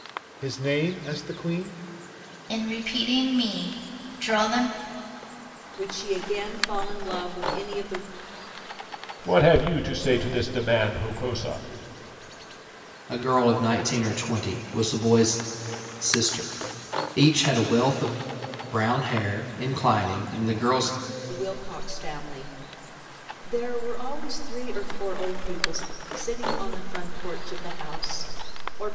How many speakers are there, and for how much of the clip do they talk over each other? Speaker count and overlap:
5, no overlap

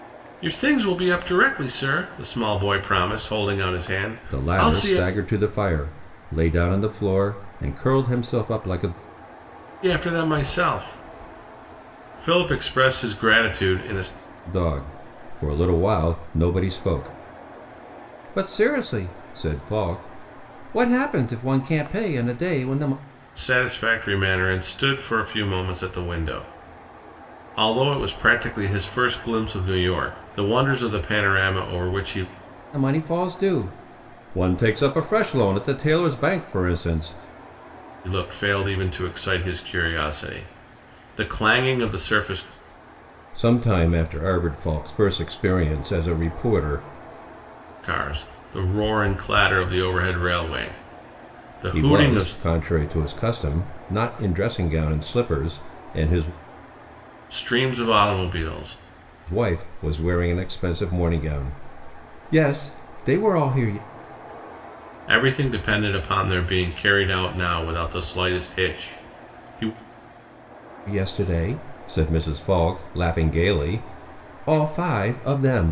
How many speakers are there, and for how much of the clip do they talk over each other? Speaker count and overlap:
2, about 2%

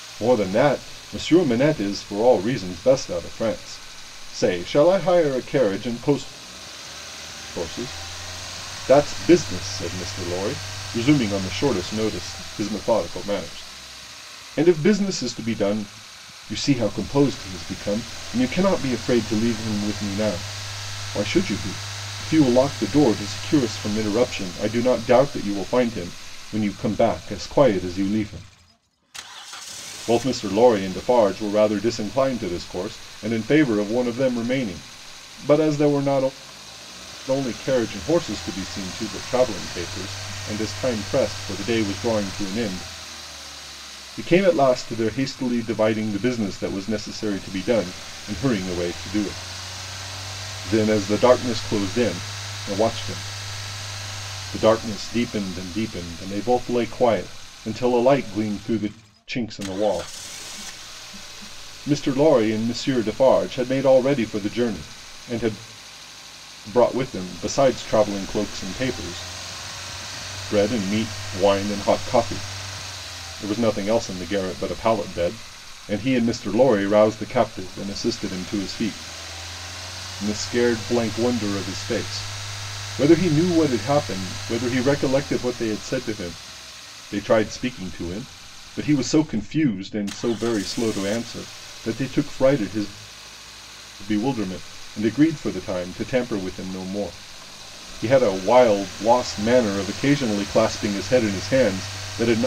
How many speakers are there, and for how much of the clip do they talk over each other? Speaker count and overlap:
1, no overlap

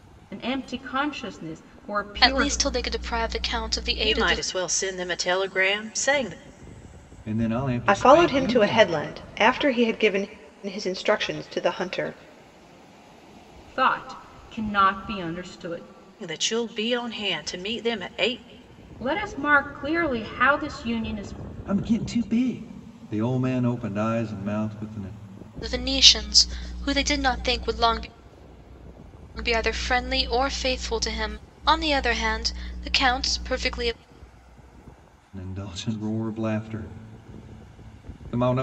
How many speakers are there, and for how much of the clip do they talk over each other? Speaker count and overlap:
5, about 5%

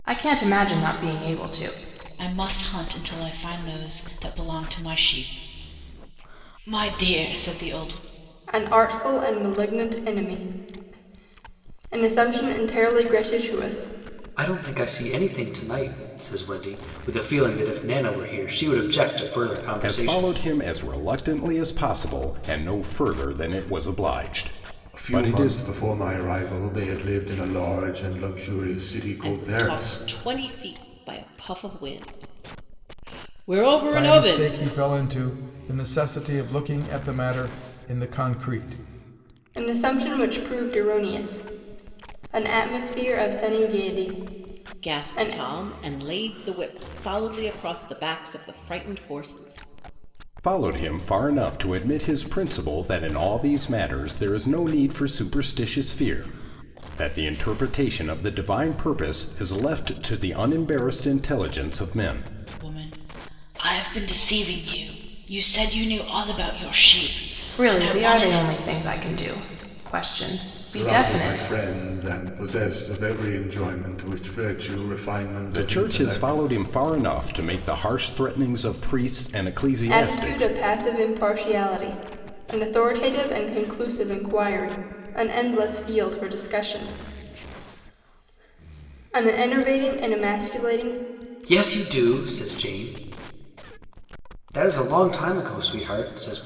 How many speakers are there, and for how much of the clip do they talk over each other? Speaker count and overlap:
8, about 7%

